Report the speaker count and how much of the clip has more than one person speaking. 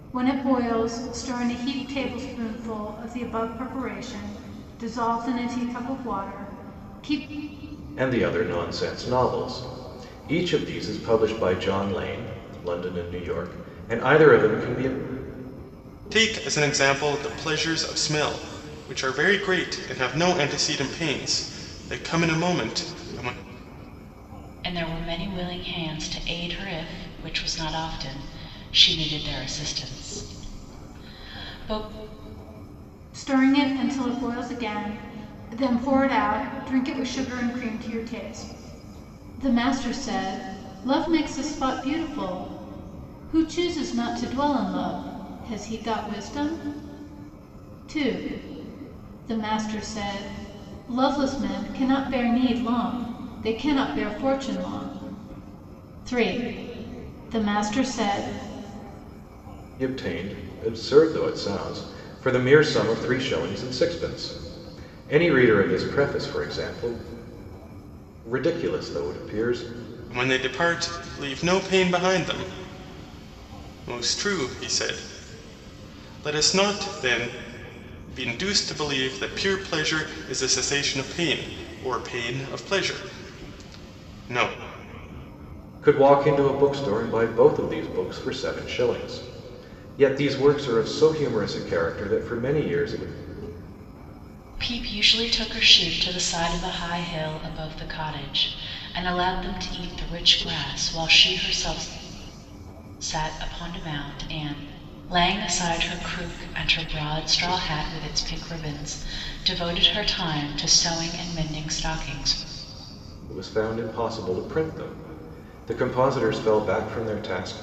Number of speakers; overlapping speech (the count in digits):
4, no overlap